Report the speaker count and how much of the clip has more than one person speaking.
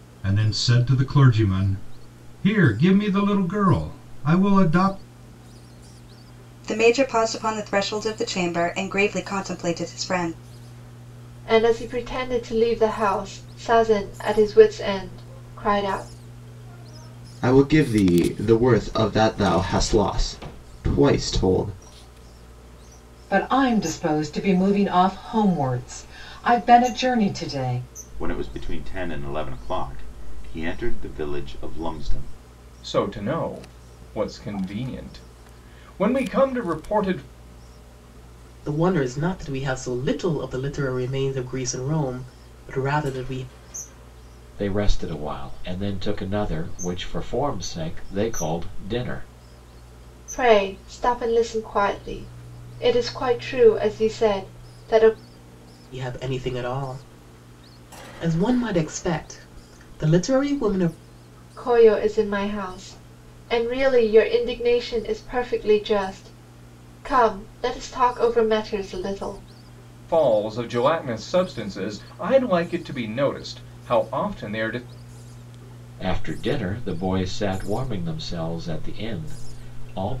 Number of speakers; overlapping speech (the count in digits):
9, no overlap